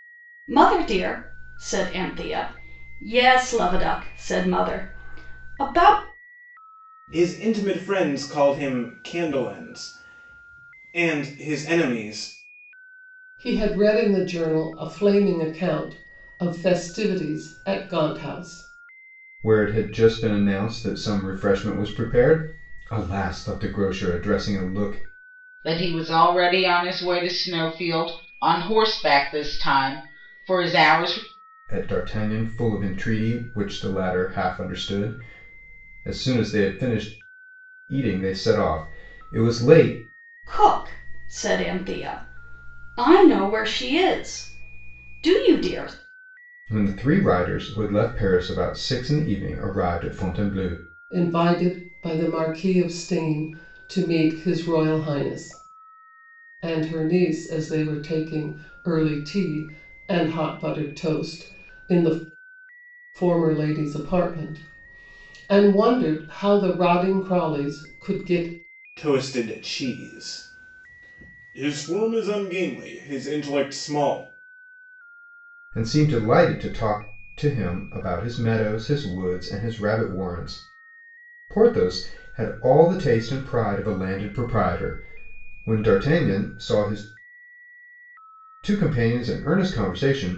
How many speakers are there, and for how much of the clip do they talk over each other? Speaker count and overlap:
five, no overlap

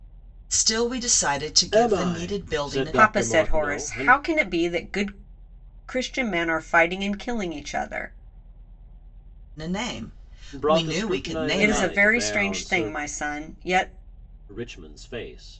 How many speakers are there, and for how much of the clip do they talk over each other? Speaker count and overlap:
three, about 31%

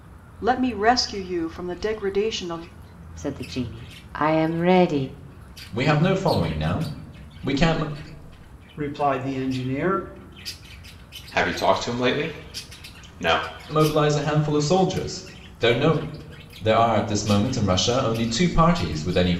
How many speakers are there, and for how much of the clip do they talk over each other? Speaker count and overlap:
five, no overlap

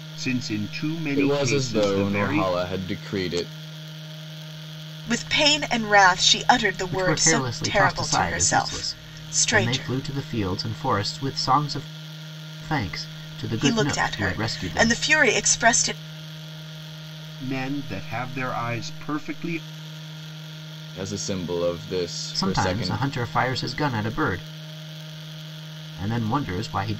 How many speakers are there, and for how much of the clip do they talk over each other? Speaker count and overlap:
four, about 23%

